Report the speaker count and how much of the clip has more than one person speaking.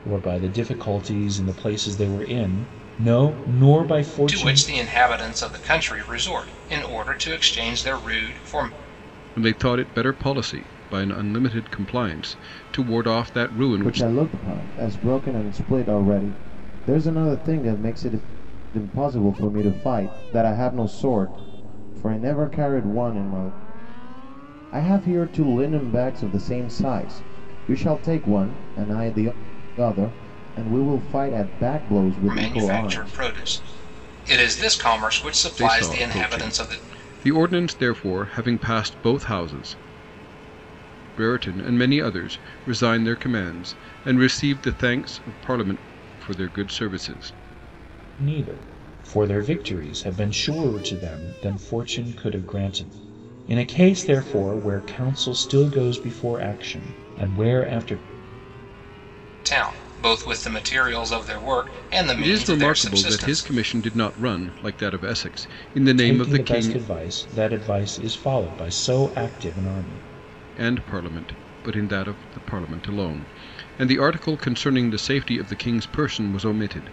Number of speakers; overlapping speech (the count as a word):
four, about 7%